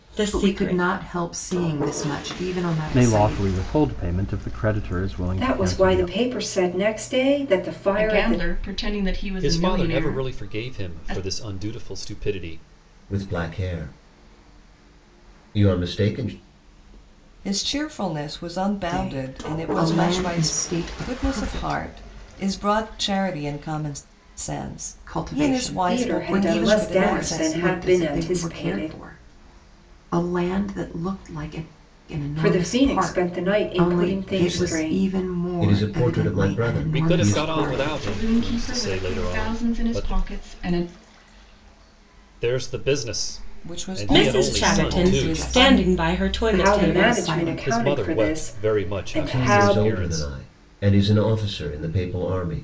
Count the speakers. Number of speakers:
eight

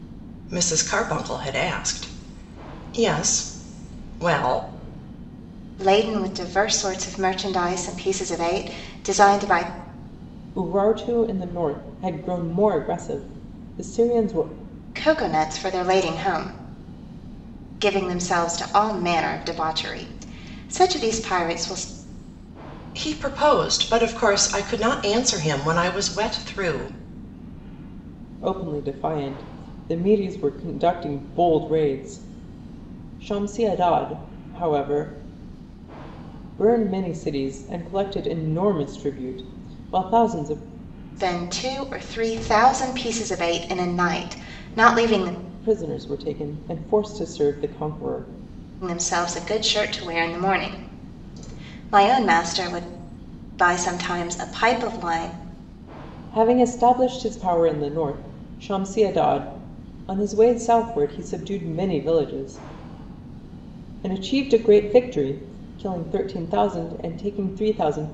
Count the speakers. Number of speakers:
three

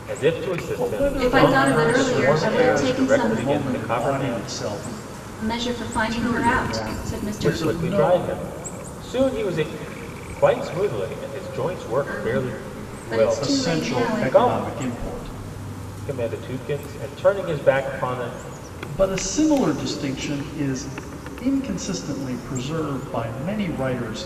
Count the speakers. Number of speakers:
three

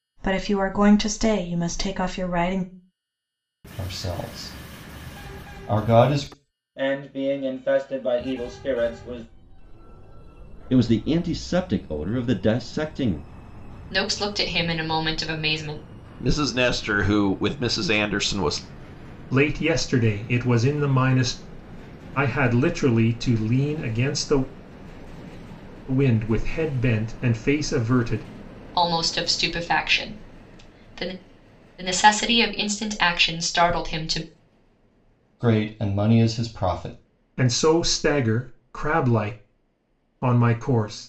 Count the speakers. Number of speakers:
seven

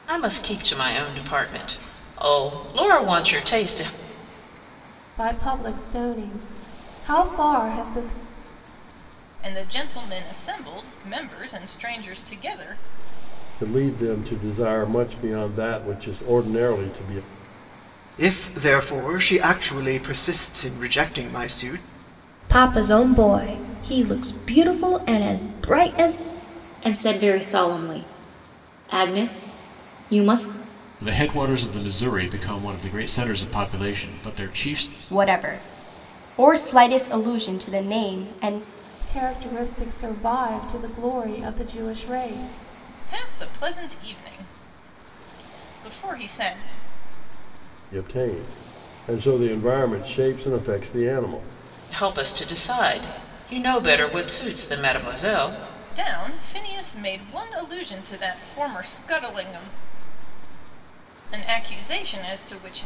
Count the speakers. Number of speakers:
nine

